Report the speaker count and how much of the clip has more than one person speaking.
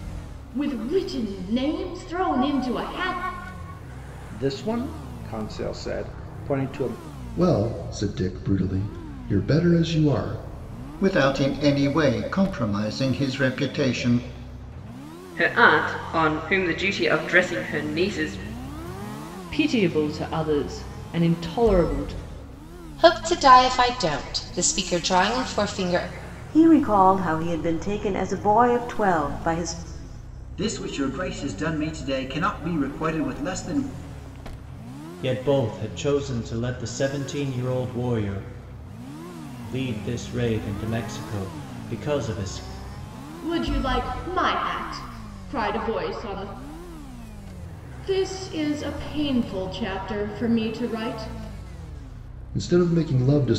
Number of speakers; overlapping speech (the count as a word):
ten, no overlap